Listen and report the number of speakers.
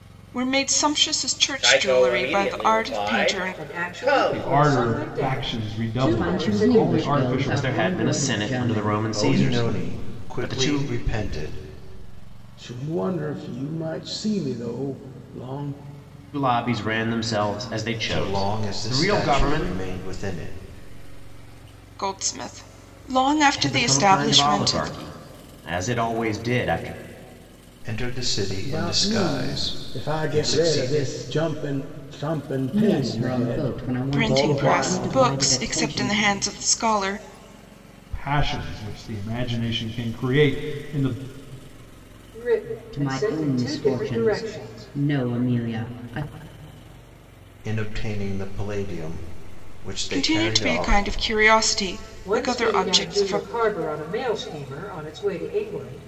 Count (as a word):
eight